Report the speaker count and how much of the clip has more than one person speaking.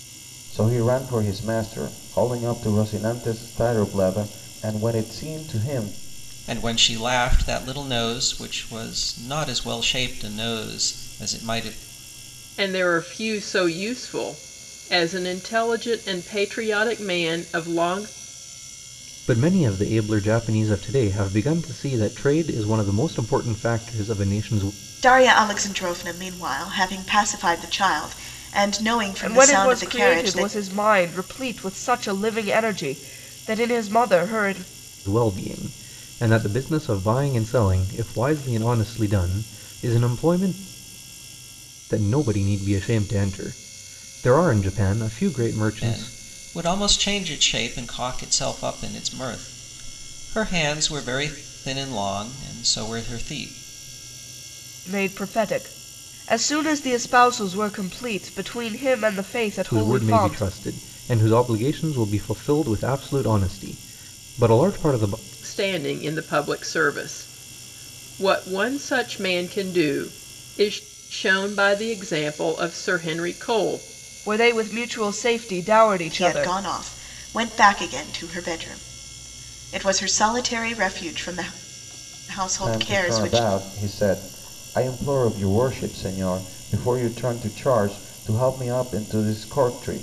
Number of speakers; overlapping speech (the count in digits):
6, about 5%